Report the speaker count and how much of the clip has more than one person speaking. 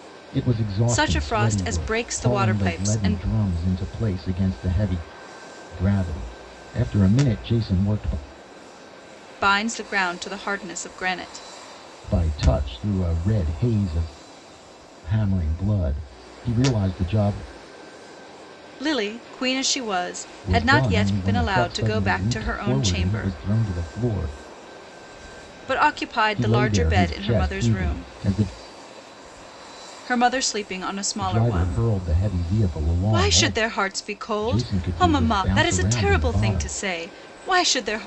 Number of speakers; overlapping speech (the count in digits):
2, about 28%